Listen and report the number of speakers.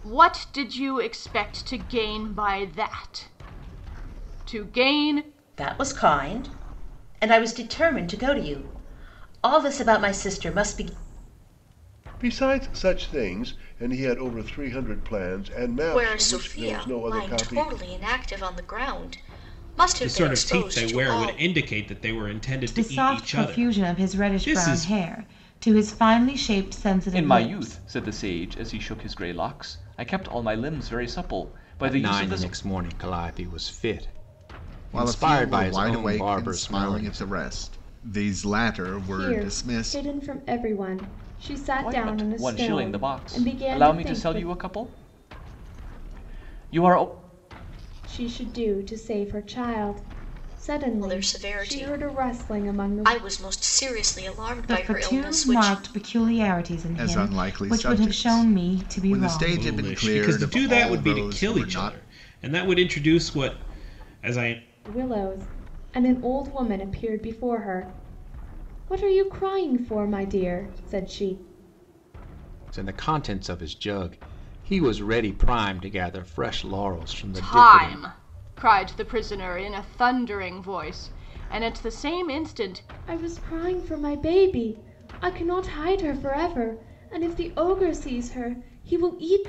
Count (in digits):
10